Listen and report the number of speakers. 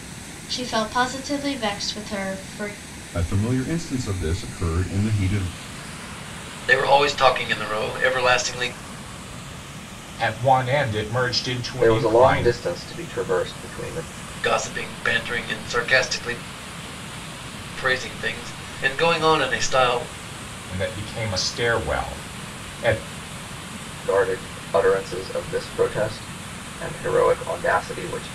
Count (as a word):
five